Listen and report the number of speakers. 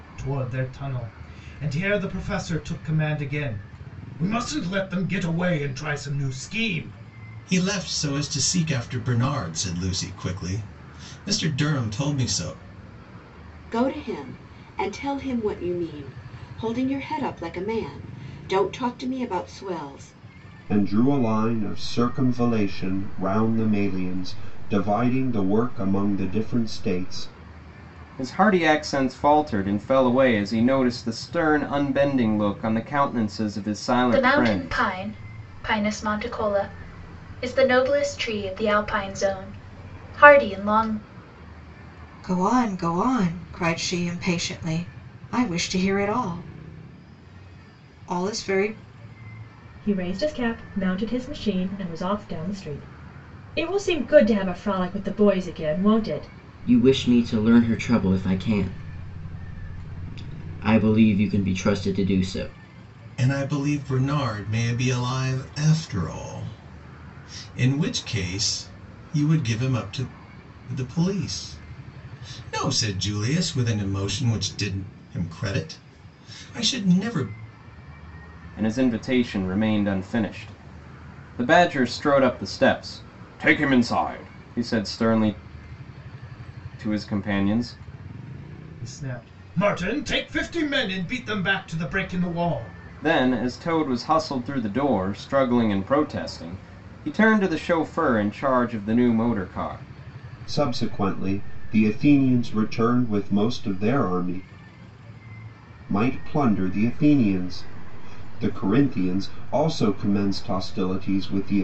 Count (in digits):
9